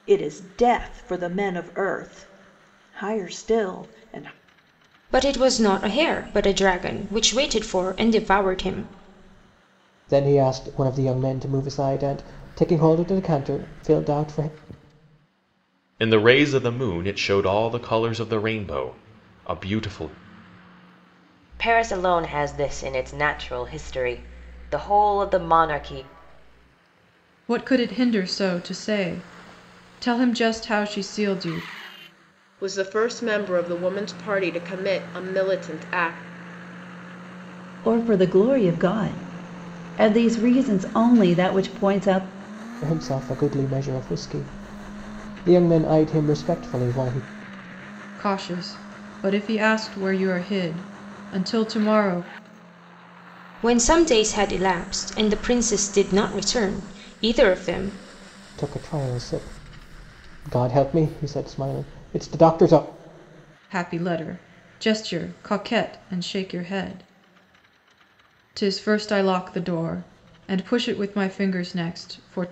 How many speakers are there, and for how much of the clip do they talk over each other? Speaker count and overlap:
8, no overlap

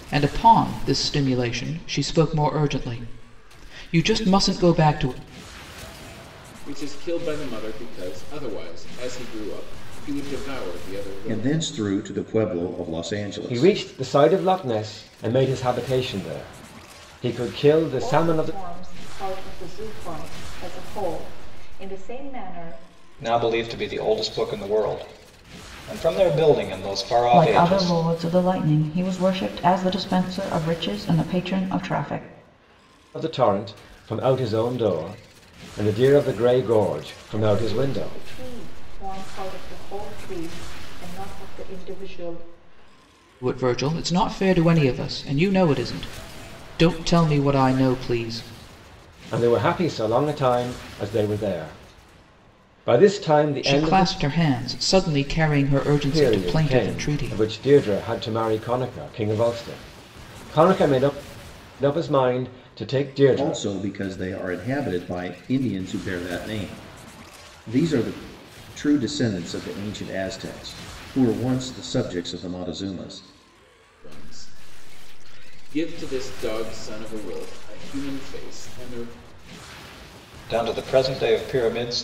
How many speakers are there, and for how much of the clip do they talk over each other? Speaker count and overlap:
7, about 6%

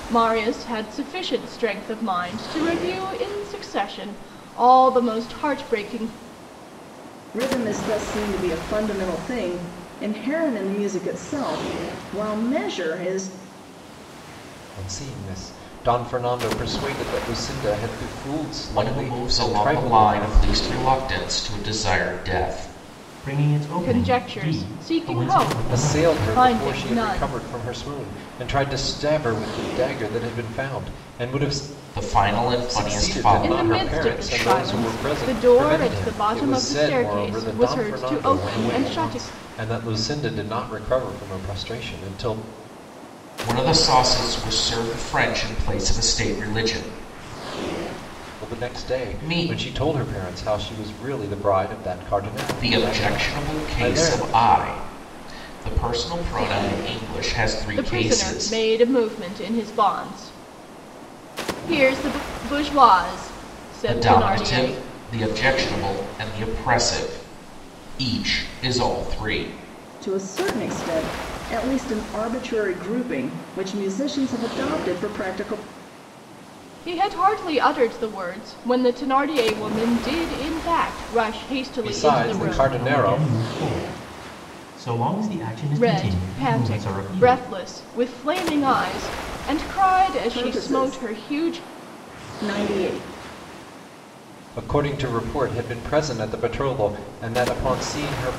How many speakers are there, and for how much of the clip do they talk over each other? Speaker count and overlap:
5, about 23%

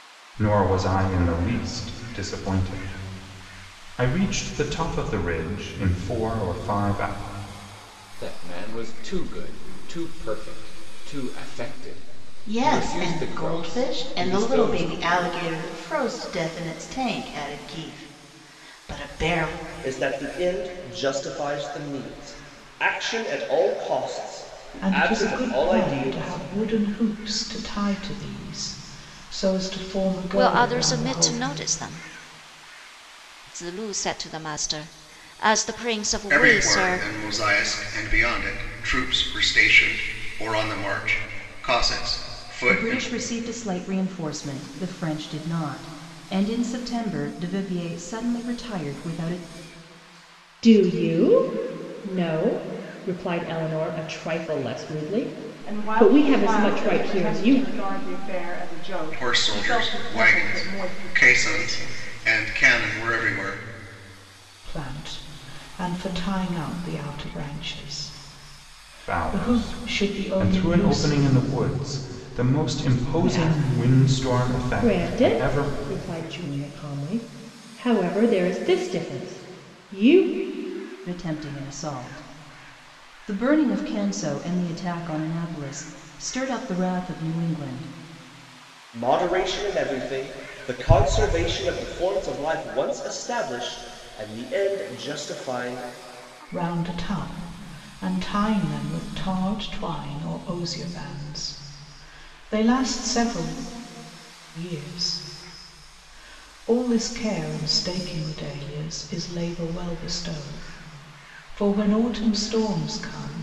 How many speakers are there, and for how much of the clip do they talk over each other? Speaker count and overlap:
10, about 14%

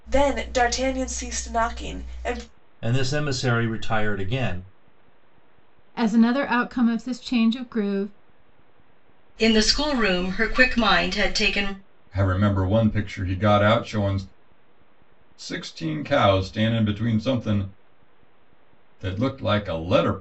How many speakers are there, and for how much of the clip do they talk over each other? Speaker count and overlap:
5, no overlap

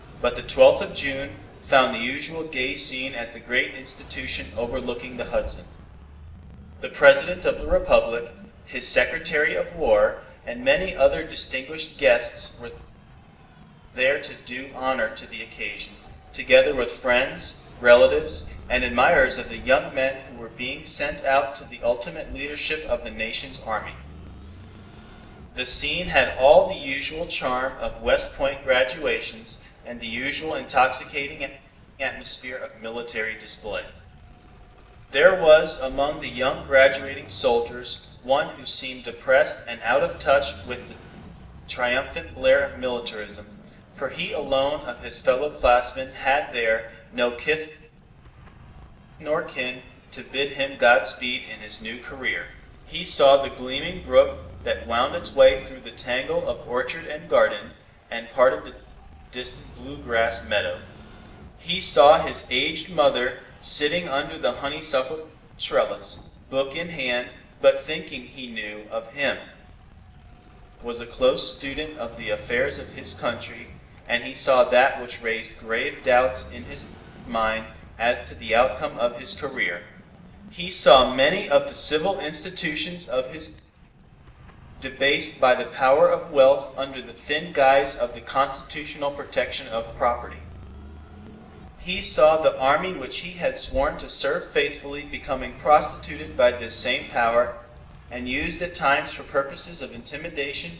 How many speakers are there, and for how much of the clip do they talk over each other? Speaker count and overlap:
1, no overlap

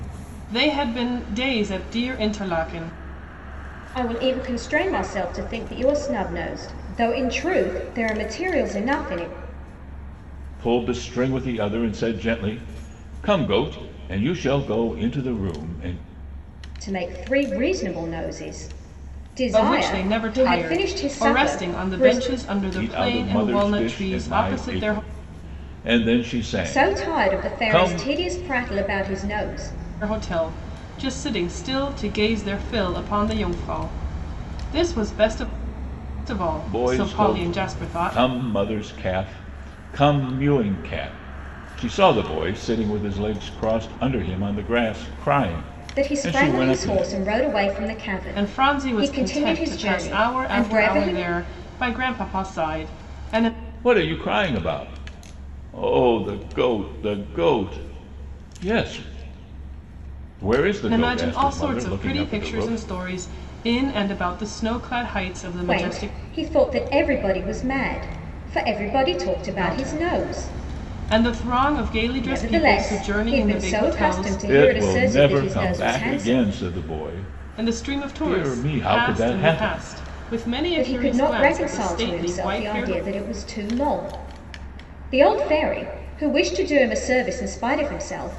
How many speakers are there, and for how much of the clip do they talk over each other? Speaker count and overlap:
3, about 28%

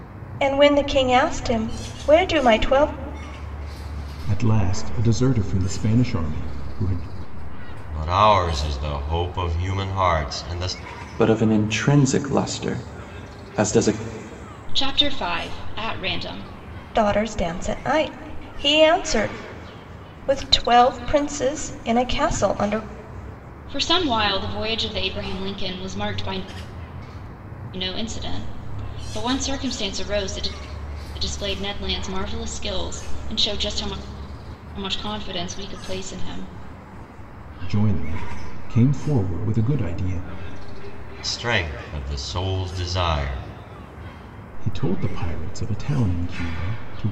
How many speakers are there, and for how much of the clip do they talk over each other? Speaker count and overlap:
5, no overlap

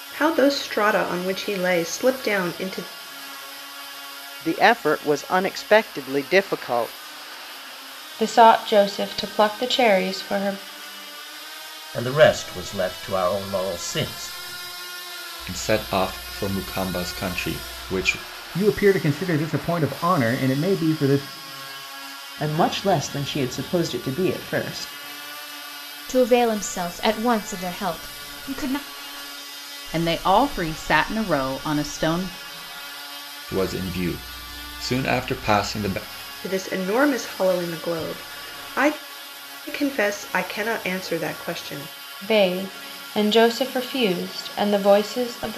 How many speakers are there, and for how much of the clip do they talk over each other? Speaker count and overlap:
9, no overlap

